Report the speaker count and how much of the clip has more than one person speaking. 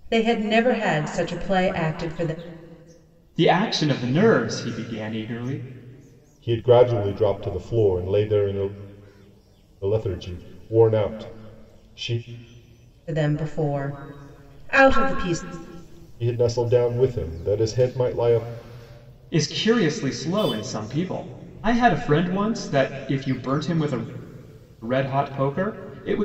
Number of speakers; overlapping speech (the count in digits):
3, no overlap